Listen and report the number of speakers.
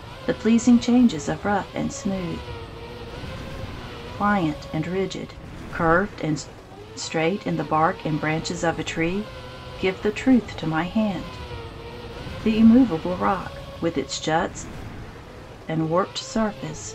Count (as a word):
one